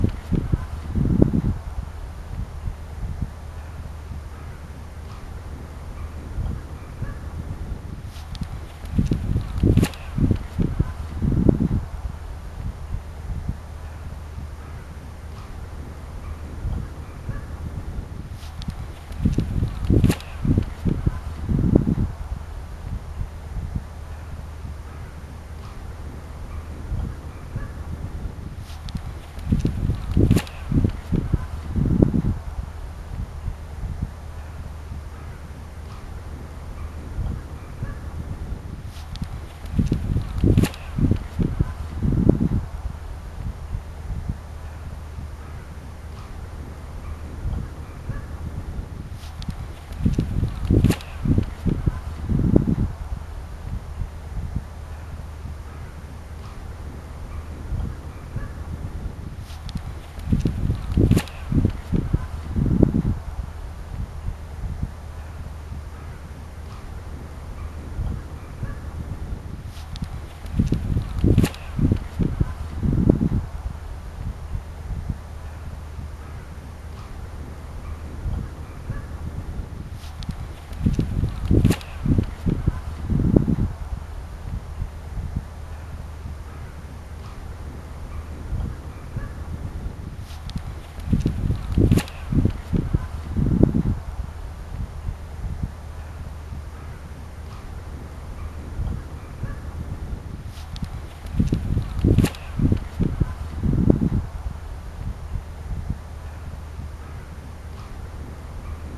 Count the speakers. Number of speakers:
0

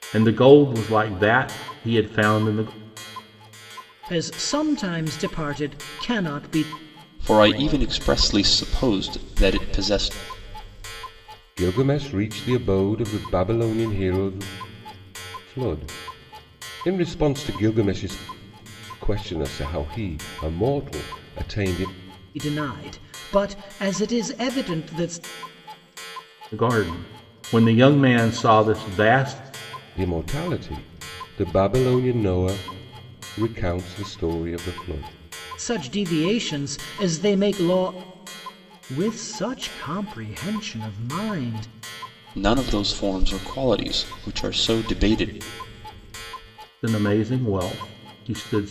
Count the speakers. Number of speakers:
4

